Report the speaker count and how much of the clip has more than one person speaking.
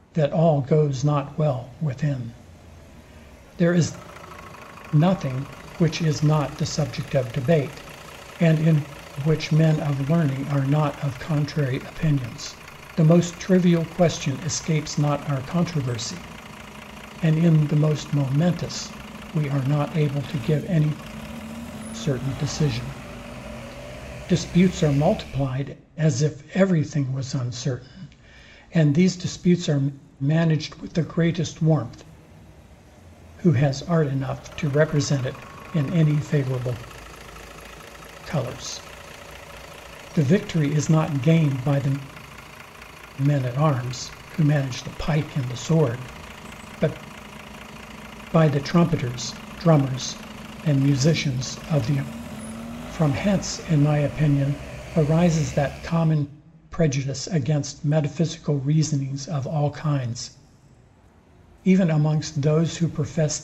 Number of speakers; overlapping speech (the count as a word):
one, no overlap